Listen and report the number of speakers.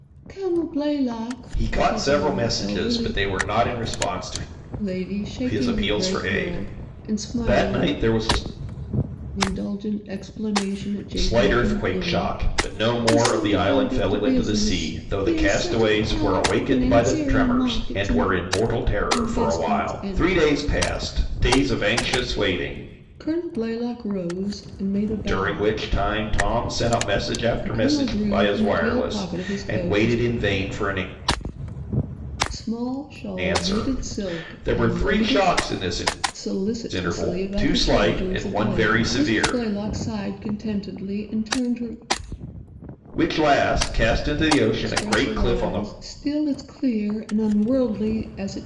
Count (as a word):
two